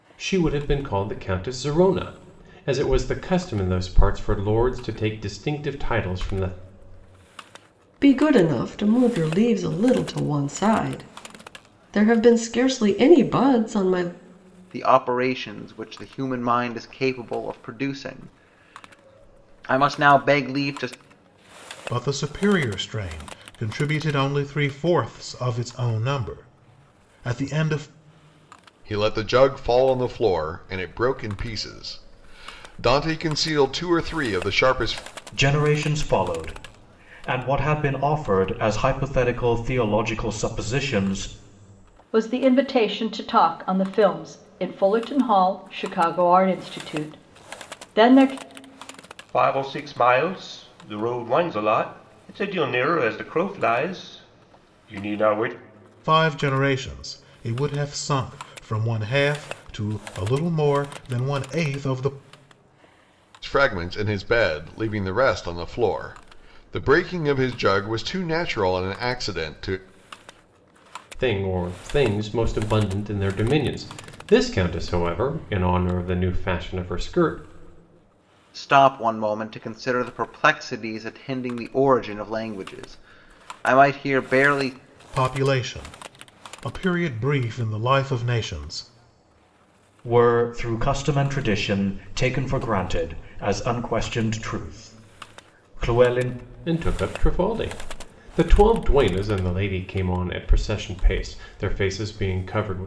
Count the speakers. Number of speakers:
eight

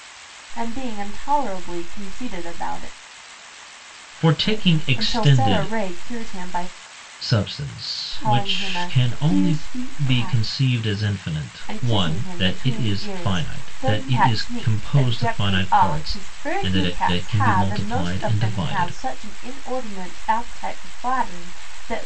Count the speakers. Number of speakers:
two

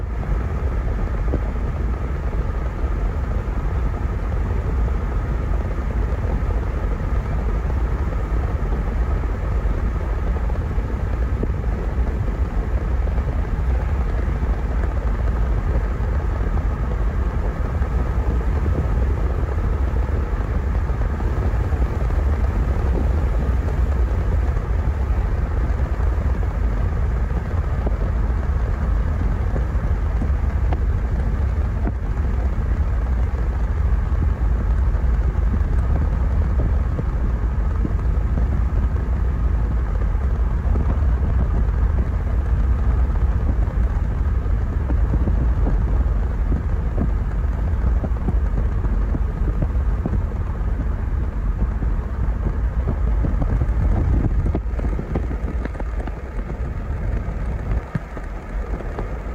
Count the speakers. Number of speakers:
zero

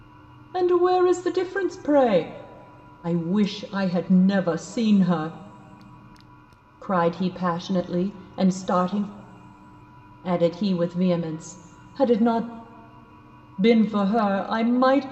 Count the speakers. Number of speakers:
one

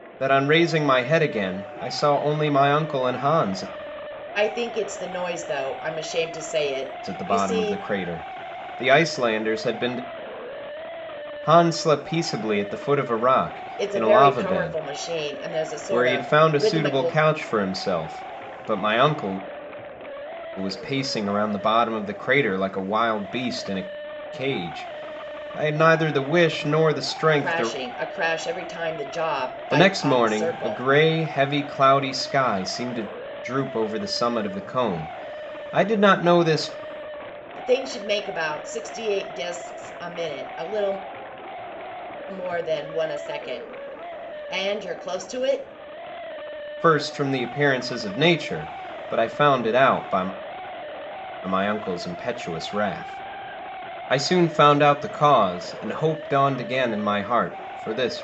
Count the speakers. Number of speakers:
two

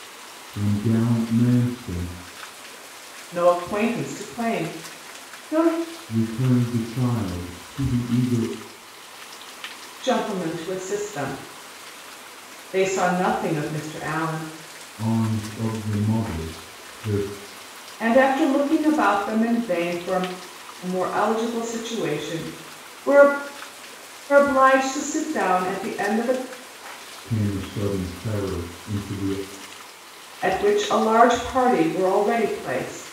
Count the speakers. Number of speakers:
two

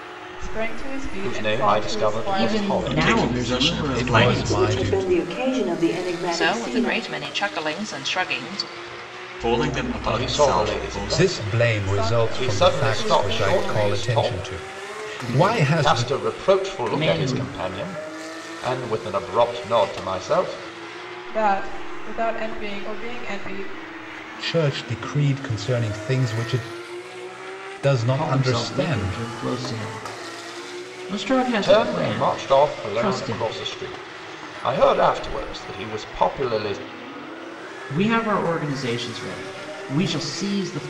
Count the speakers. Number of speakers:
seven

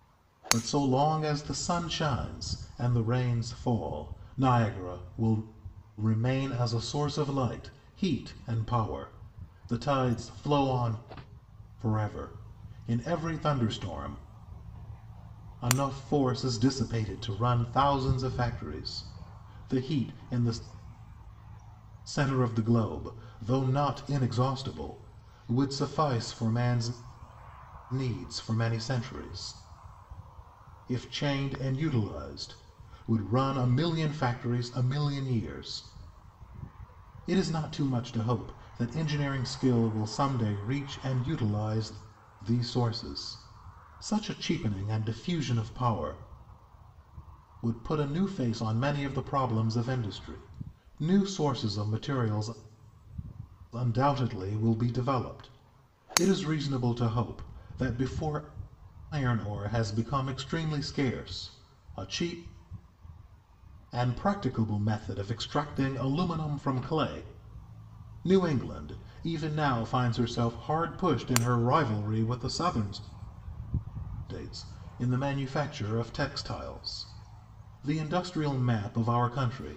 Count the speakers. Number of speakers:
one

